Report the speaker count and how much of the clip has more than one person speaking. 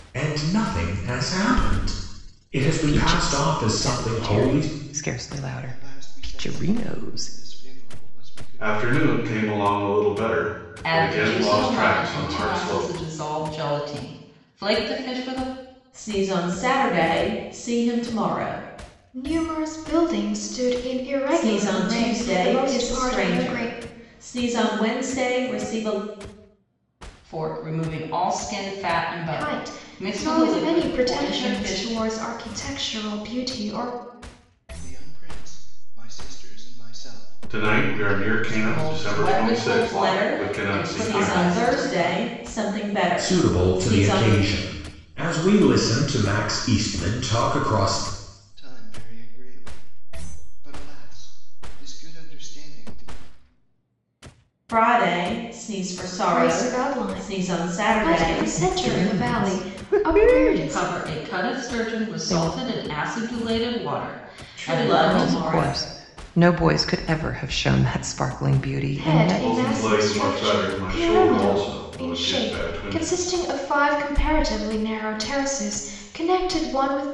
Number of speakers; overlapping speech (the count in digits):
7, about 38%